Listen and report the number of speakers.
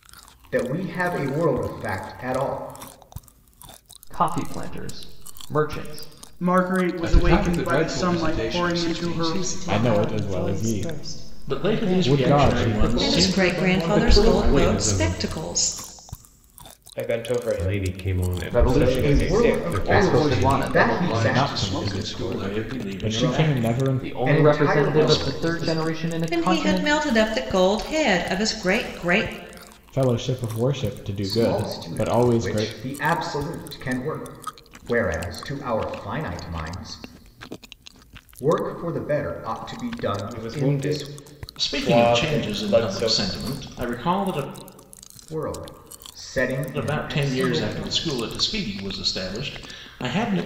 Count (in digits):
10